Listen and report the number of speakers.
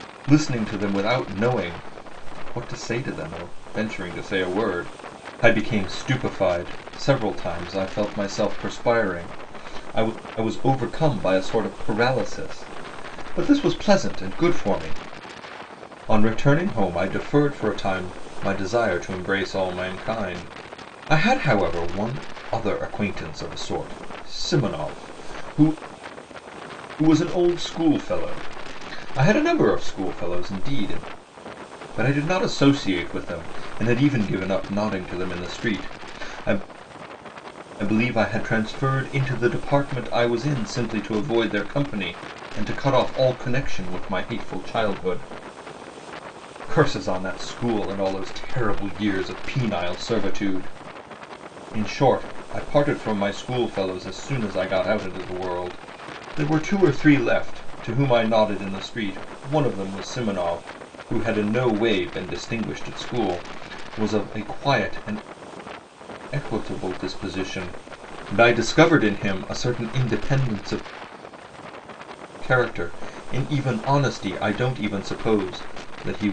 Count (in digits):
1